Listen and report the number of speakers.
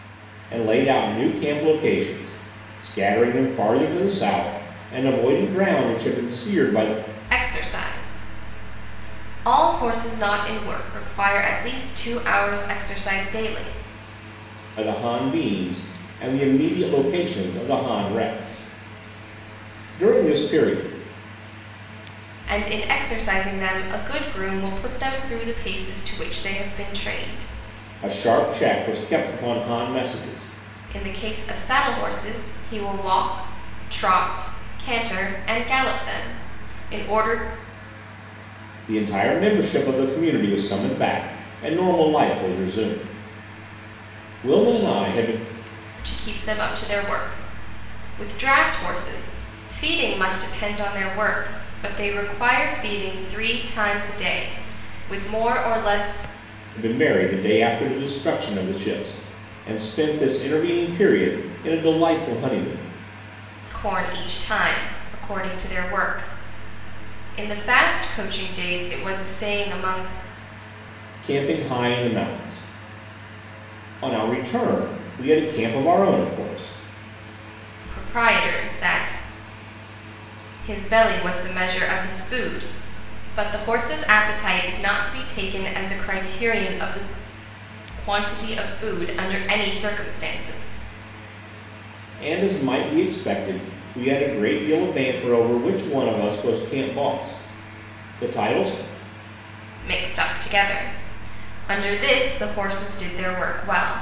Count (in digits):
2